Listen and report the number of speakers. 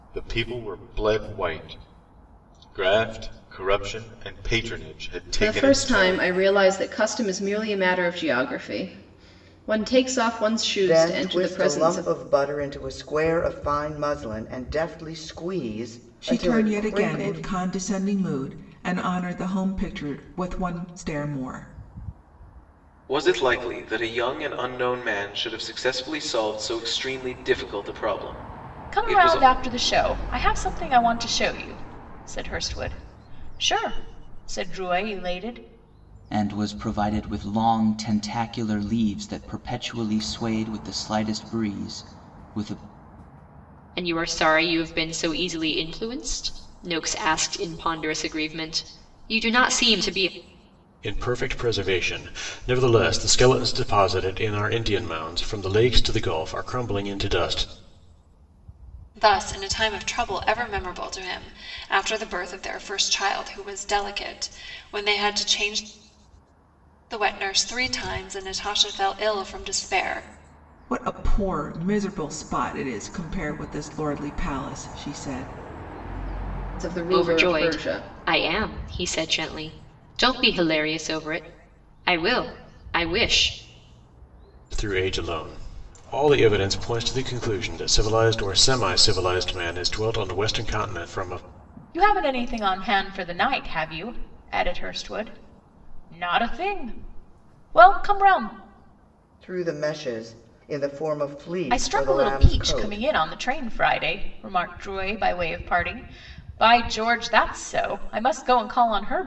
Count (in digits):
10